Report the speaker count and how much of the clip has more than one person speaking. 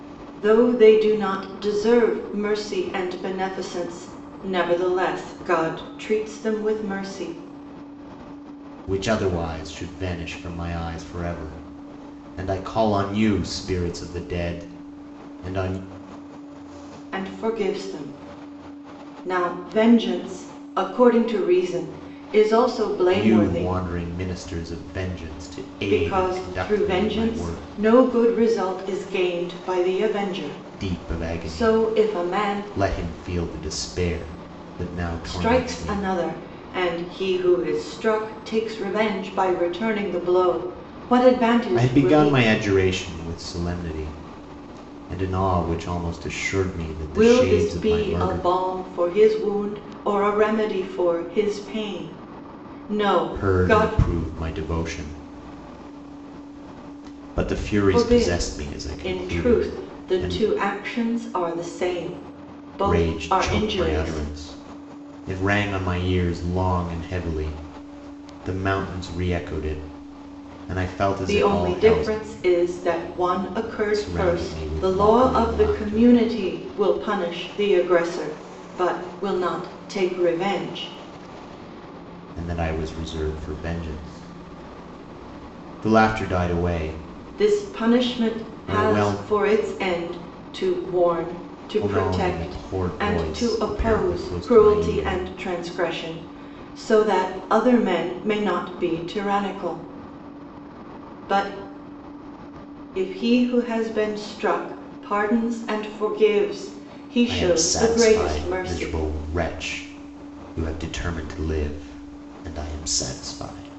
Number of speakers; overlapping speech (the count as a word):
two, about 19%